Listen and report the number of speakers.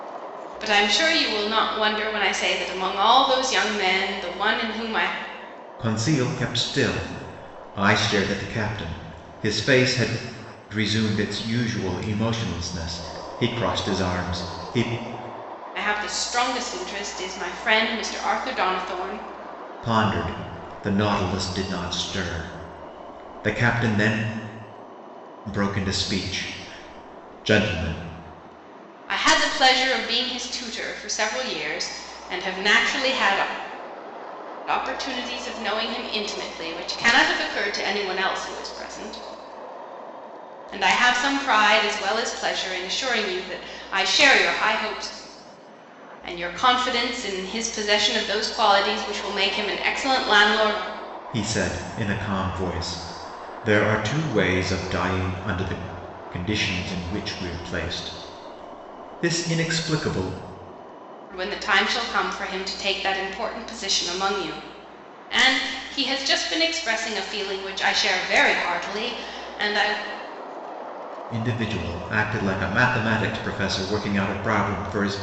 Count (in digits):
2